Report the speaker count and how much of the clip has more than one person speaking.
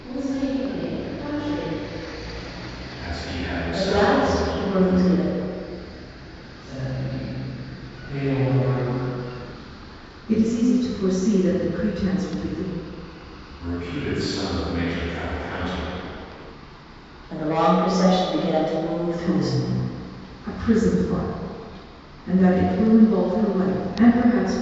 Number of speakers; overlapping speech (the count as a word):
five, about 7%